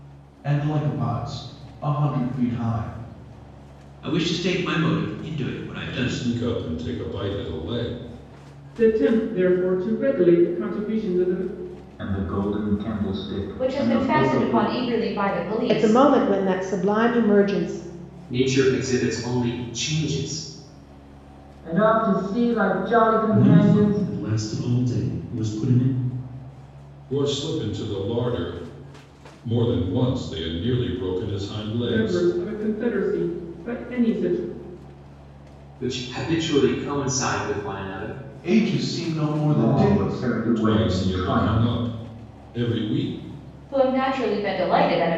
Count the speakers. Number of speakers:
10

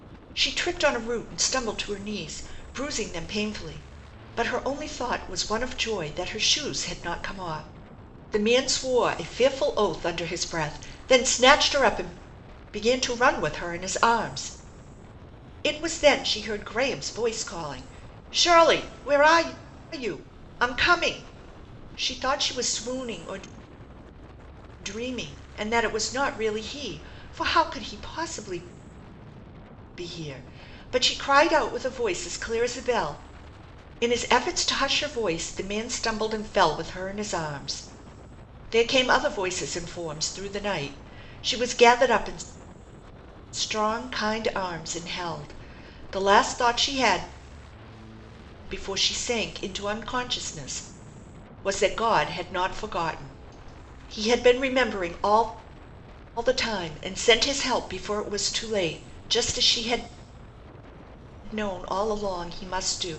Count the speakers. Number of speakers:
1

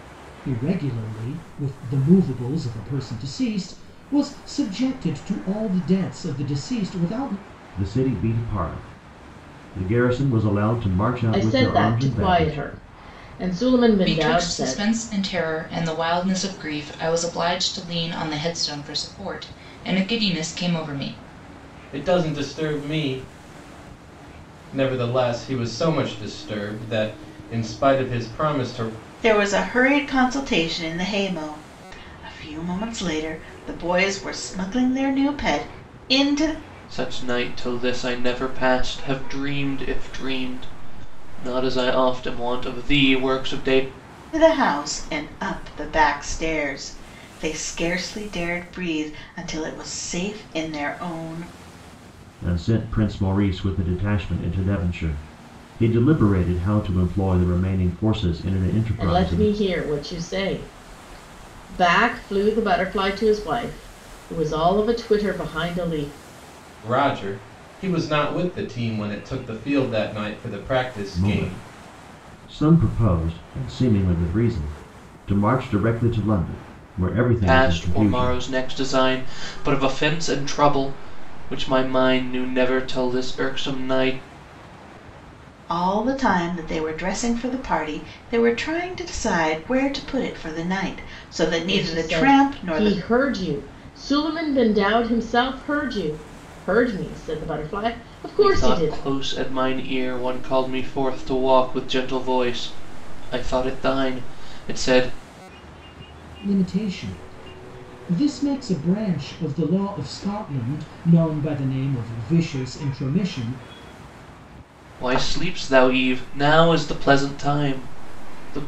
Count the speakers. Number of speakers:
7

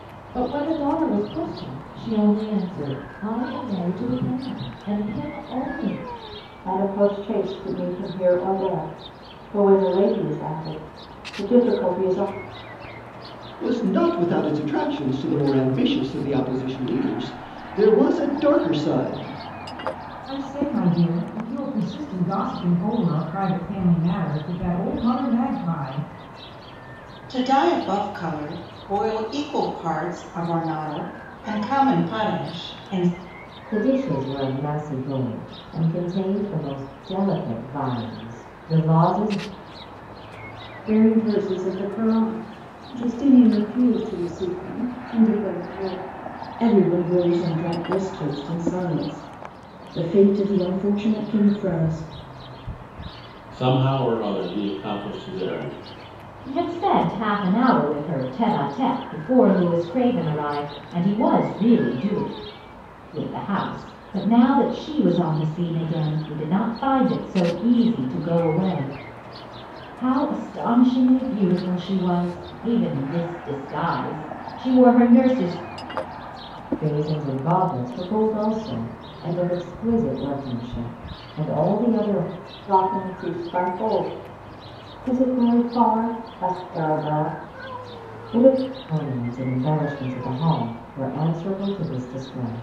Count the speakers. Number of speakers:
10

